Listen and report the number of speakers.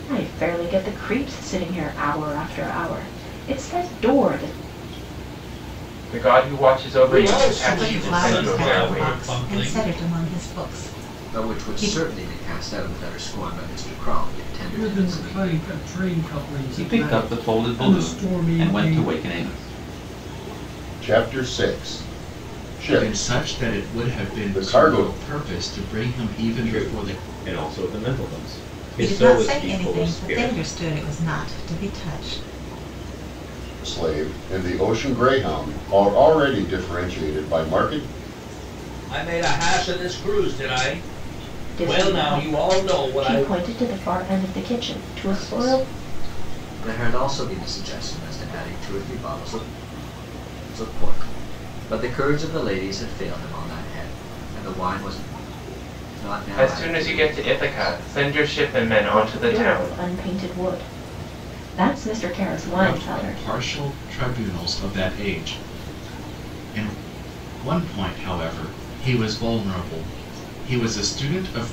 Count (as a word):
ten